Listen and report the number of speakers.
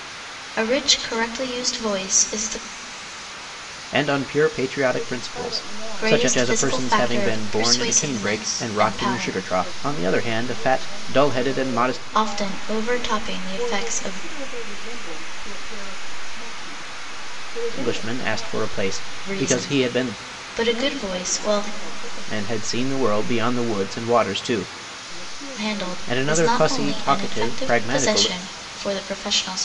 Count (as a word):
three